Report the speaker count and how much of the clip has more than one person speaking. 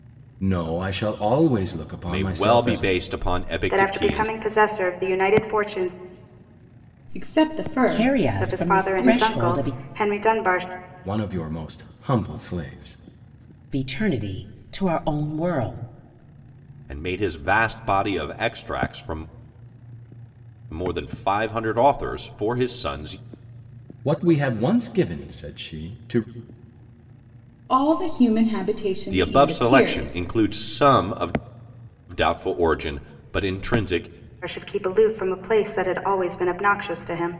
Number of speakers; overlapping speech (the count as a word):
five, about 12%